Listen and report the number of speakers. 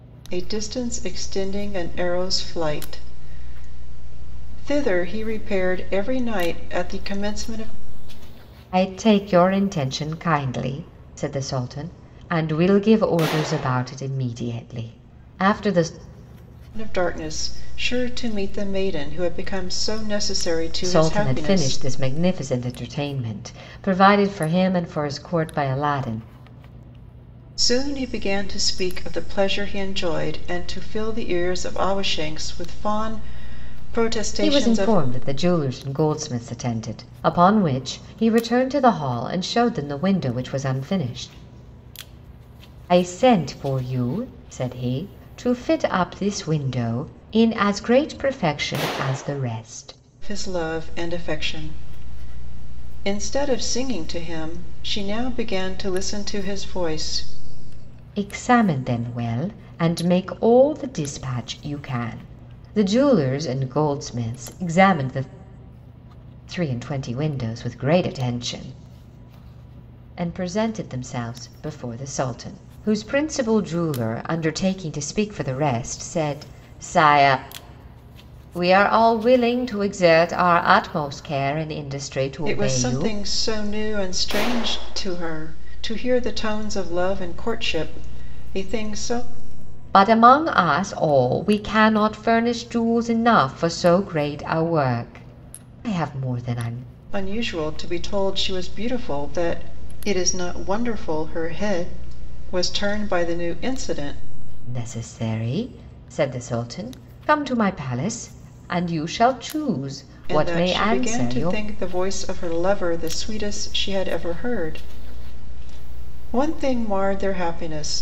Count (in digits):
2